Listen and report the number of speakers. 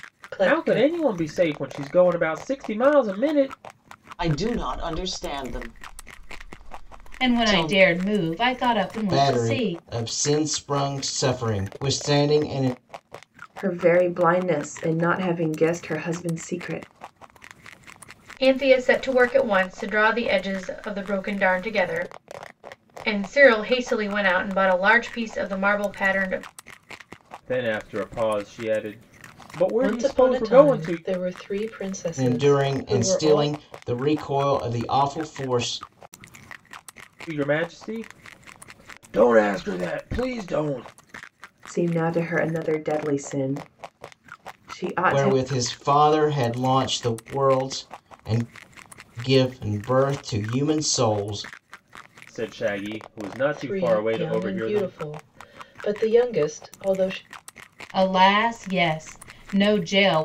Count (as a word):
seven